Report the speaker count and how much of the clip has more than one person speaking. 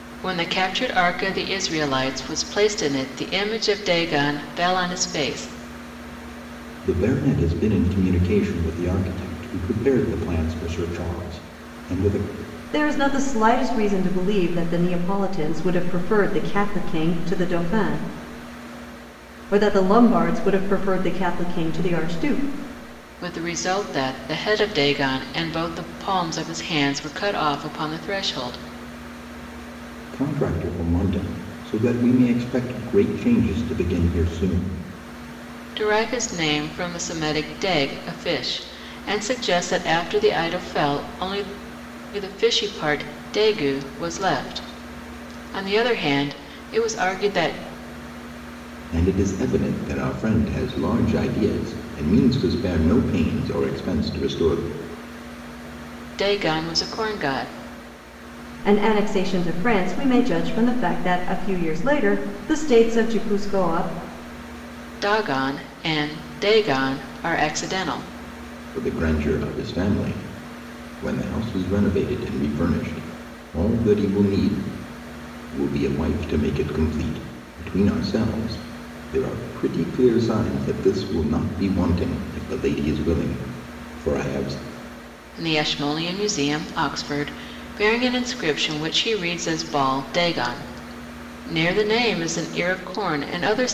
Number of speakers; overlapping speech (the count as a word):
three, no overlap